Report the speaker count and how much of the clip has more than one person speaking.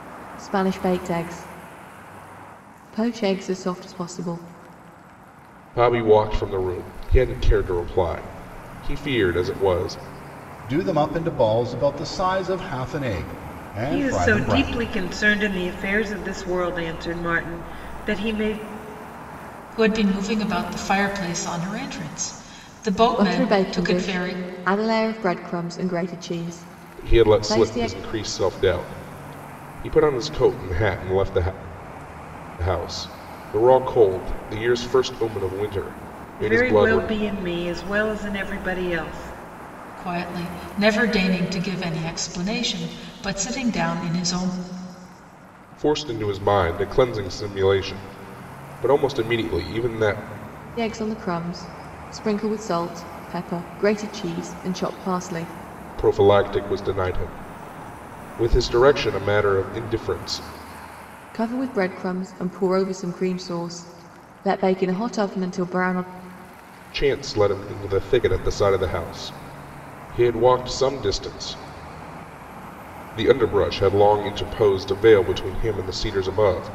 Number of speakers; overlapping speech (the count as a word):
five, about 5%